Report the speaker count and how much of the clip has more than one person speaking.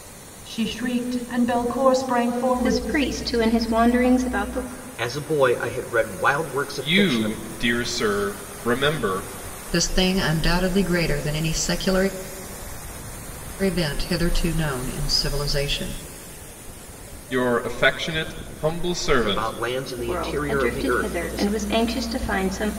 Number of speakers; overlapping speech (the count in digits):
5, about 12%